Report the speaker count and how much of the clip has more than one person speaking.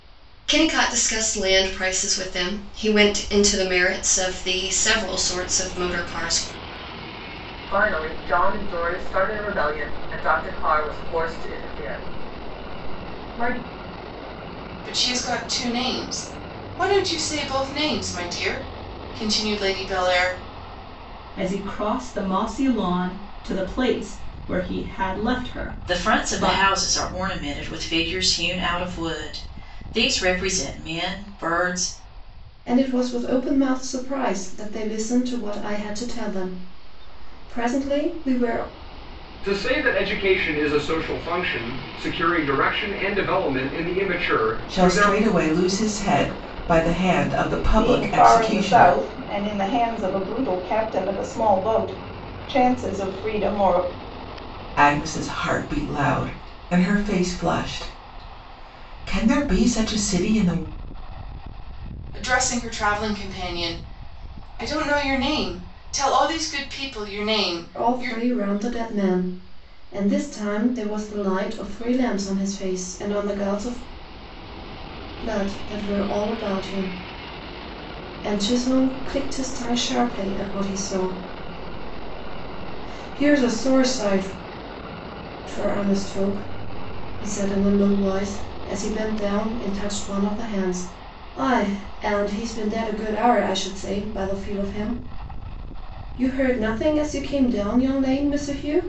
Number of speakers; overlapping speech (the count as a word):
nine, about 3%